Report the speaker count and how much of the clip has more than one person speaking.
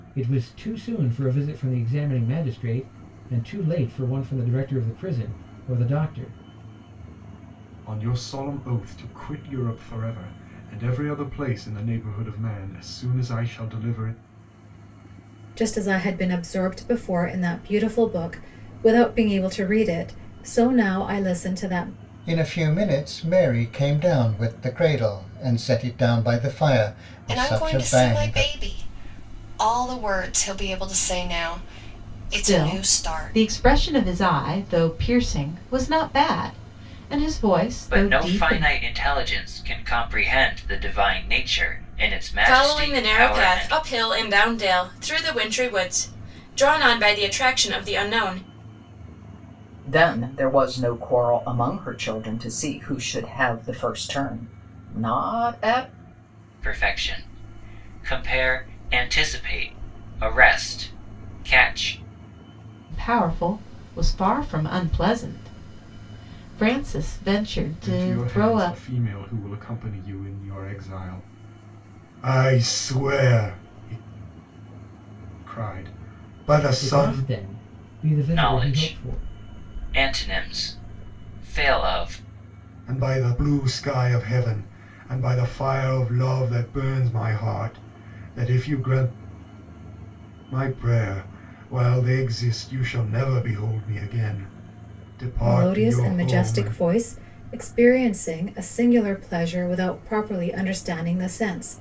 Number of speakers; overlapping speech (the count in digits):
9, about 8%